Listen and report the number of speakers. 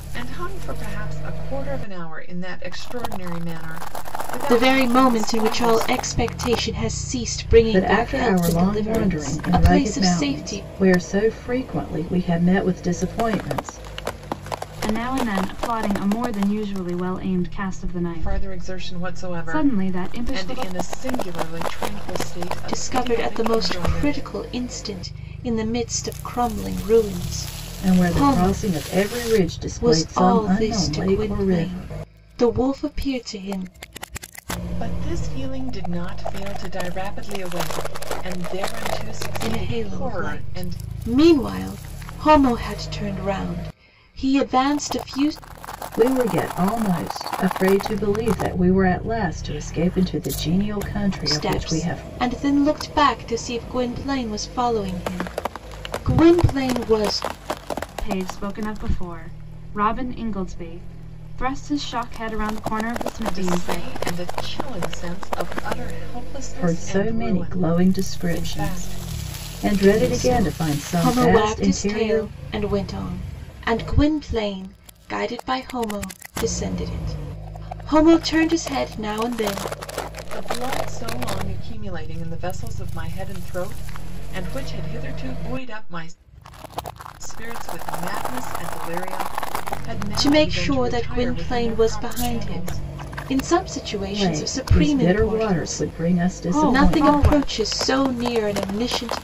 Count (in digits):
4